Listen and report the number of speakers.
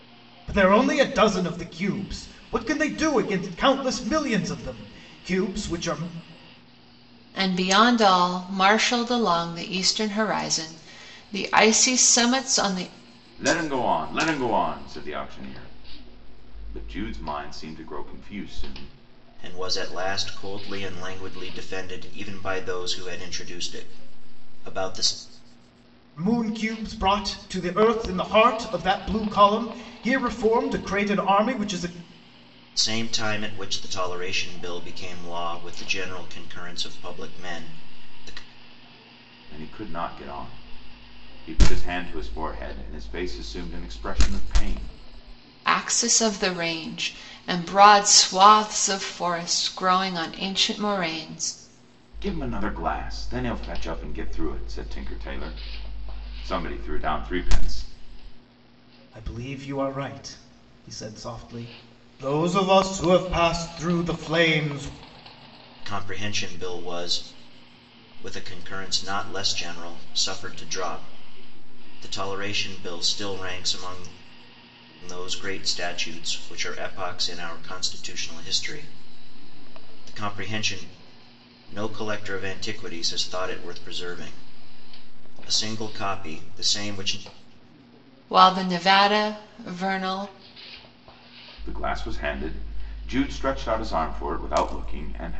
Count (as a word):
four